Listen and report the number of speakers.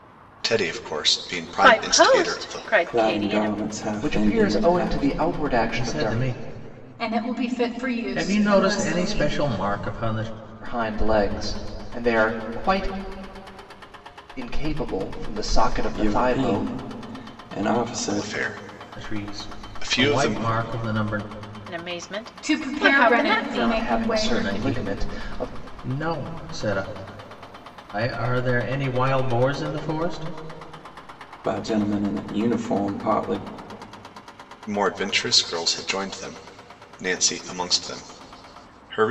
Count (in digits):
6